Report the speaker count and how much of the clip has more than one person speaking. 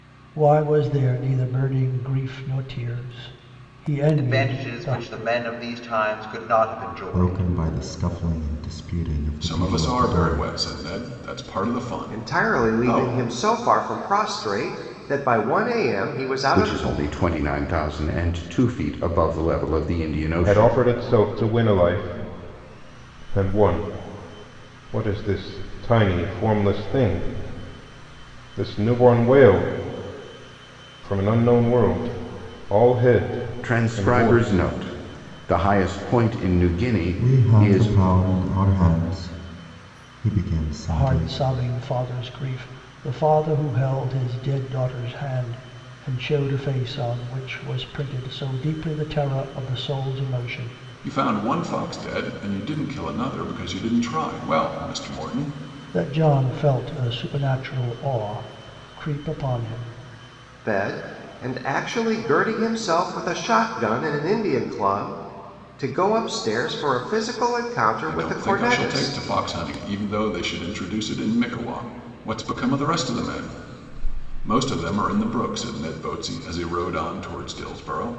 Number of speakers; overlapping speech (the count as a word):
seven, about 10%